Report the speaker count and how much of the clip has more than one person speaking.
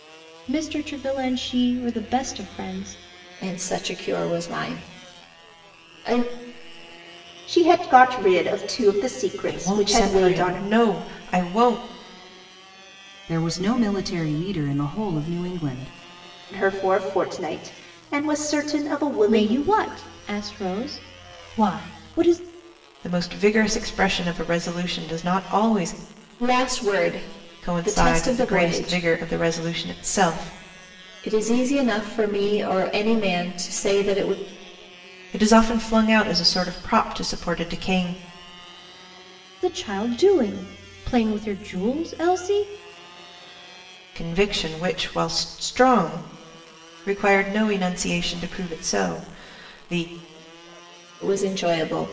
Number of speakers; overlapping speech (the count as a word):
five, about 6%